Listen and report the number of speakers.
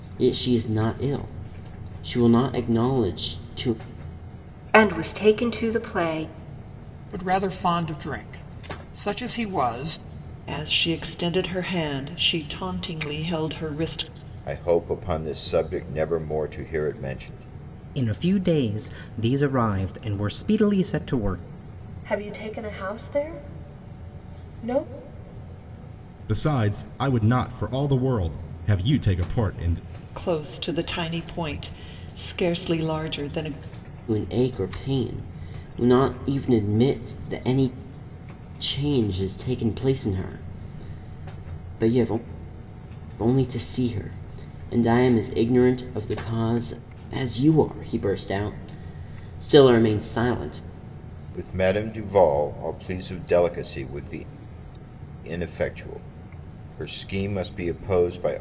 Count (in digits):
8